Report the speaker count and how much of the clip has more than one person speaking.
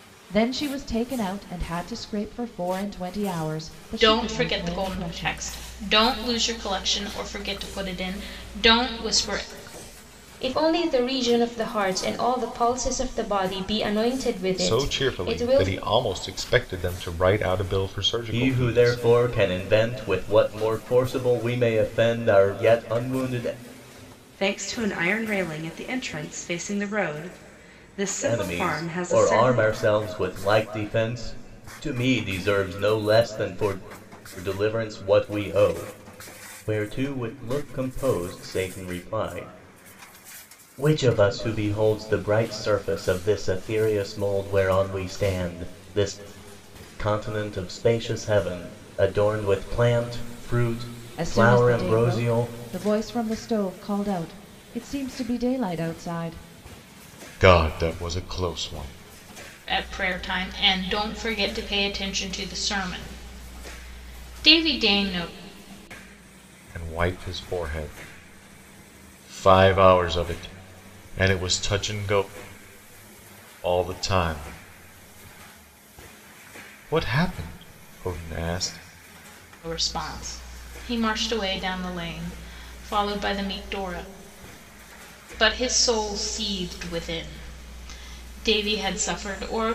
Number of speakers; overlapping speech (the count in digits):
6, about 7%